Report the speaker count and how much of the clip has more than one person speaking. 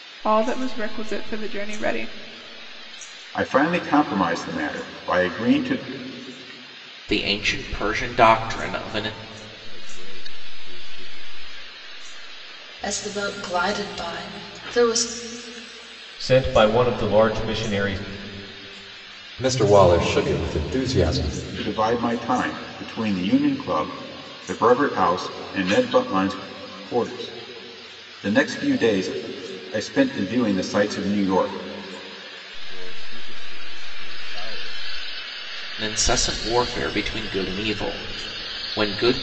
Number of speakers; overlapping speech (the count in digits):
7, no overlap